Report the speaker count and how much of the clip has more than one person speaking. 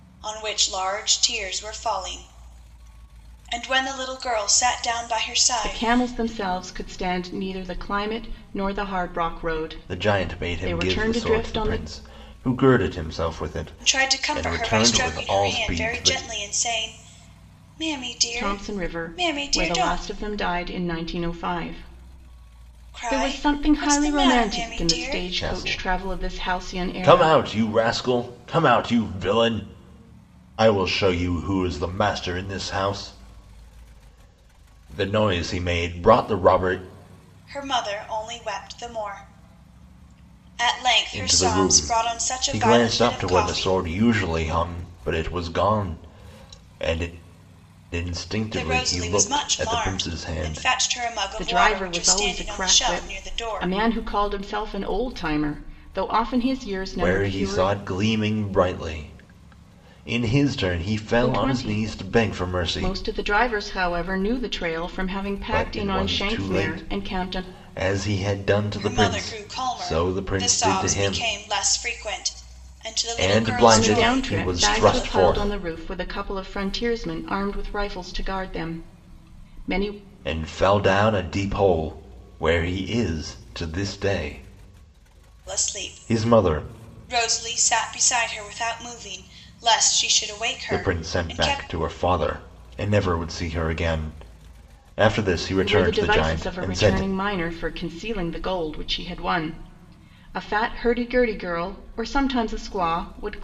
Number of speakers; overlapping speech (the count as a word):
three, about 31%